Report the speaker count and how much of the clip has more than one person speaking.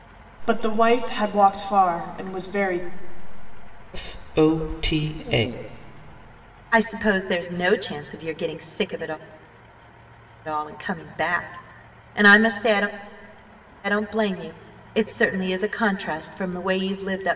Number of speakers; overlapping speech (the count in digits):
3, no overlap